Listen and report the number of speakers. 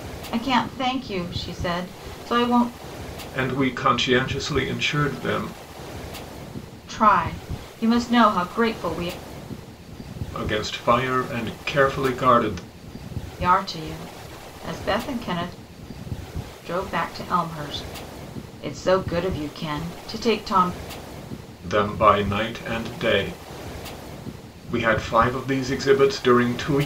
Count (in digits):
2